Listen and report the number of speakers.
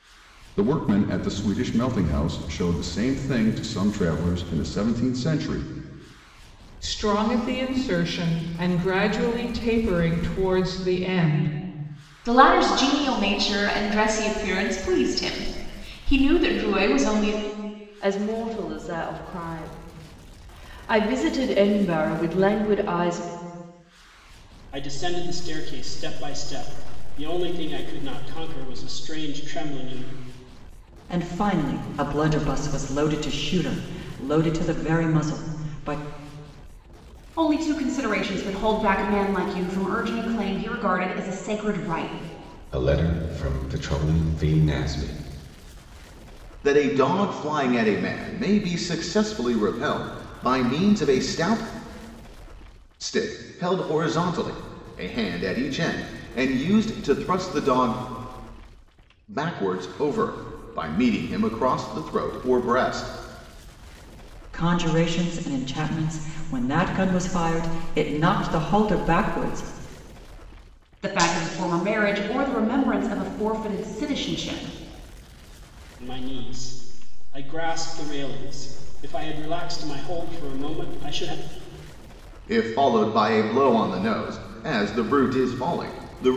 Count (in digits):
9